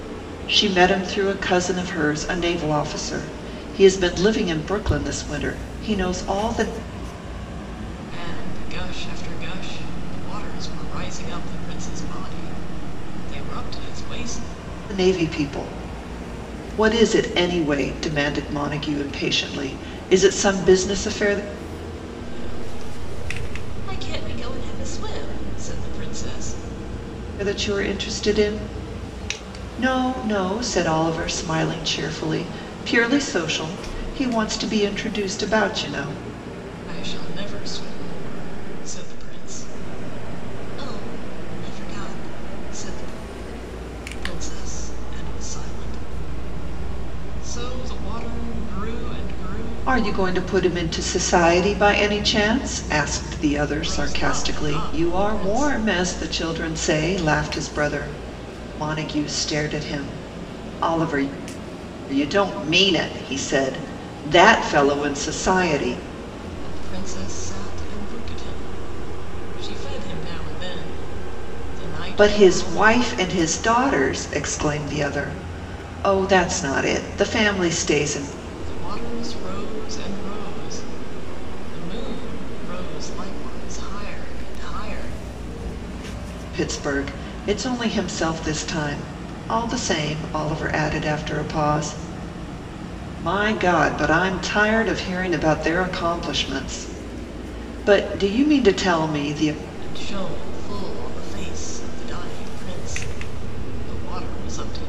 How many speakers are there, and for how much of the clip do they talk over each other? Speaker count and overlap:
2, about 3%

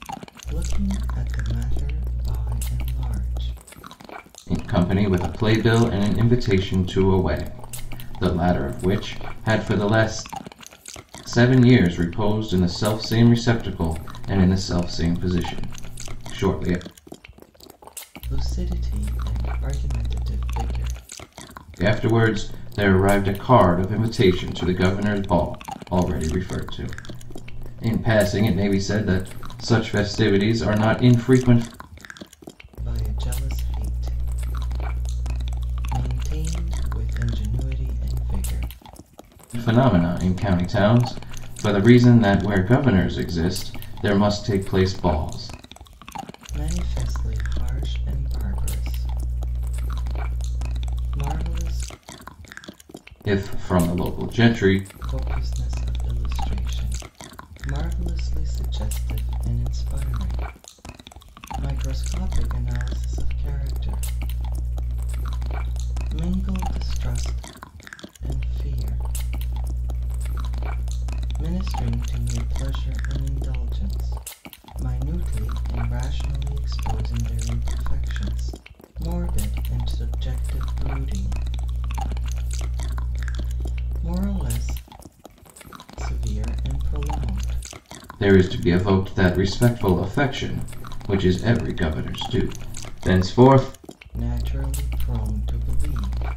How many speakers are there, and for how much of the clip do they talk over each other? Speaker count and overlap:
2, no overlap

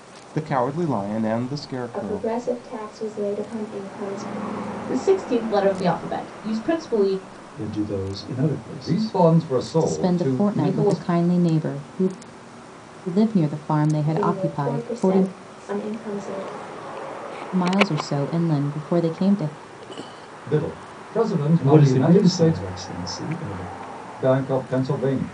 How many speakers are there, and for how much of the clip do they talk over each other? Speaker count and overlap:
6, about 18%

